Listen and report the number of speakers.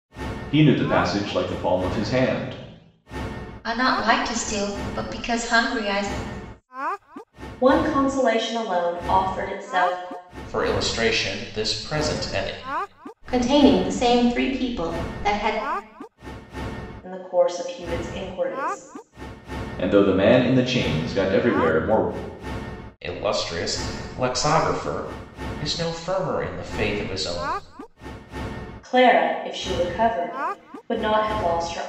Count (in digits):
5